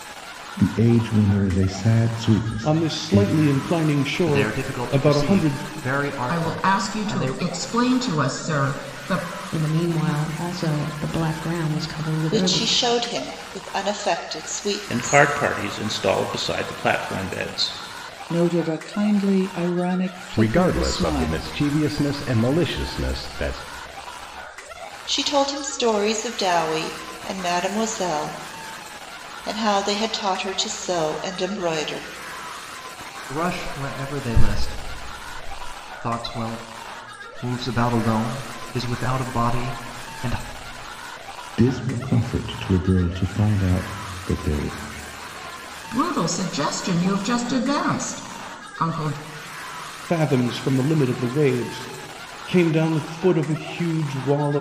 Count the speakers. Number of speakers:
nine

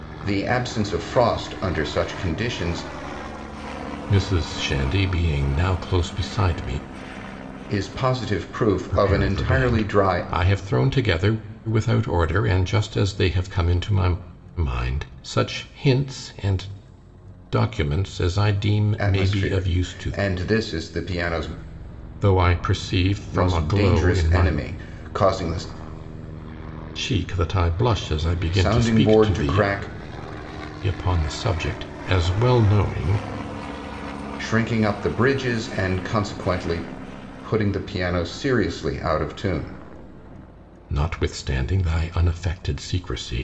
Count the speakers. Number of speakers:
two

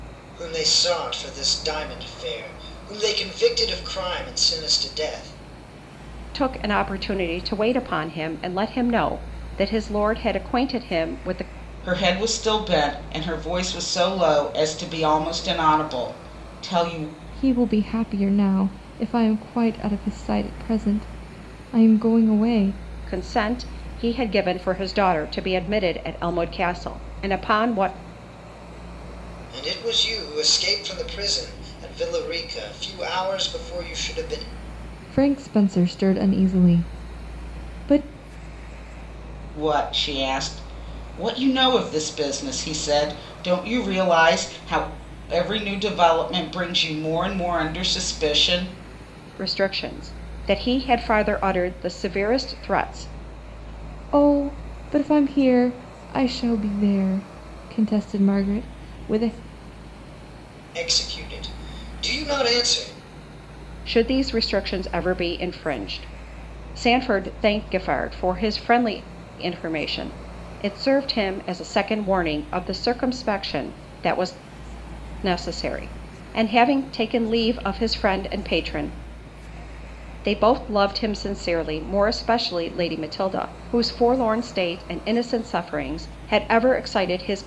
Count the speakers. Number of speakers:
four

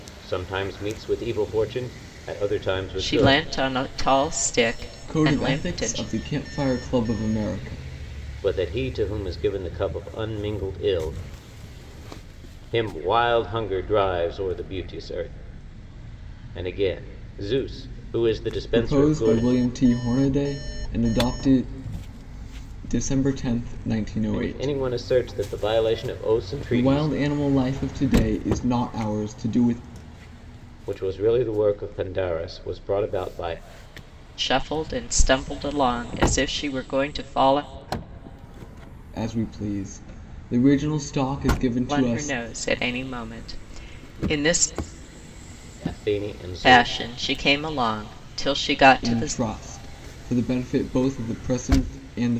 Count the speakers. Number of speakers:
three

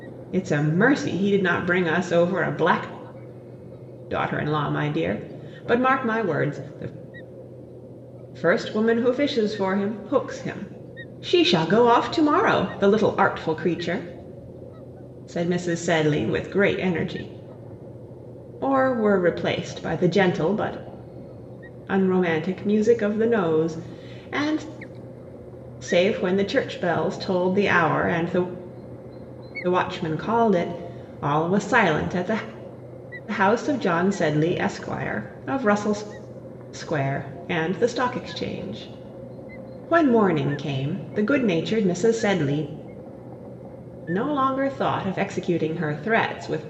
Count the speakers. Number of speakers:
one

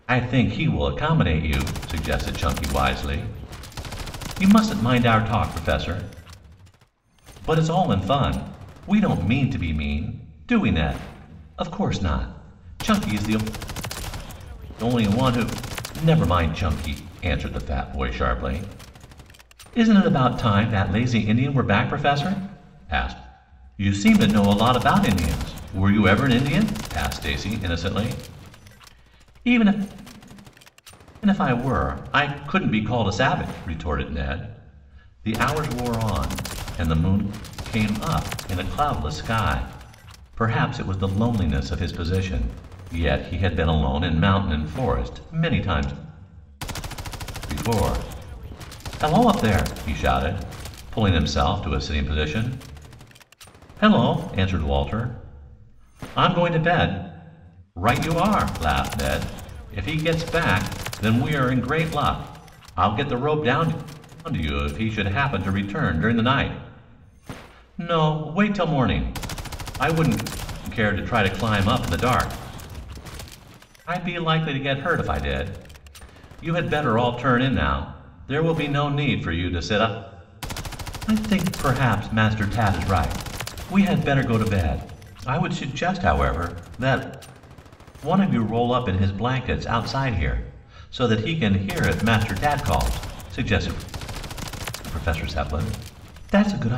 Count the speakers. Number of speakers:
one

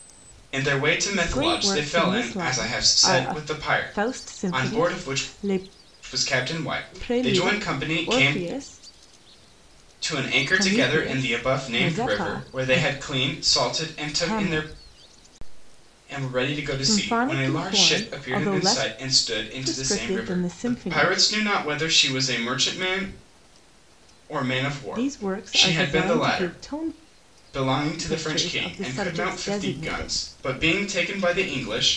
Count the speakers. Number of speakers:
two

